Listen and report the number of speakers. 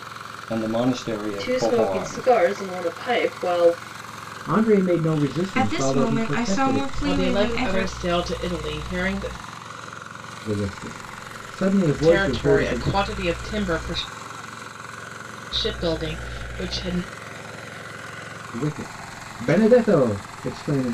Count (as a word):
five